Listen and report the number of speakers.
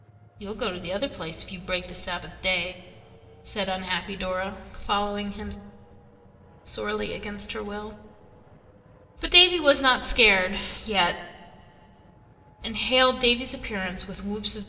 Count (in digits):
1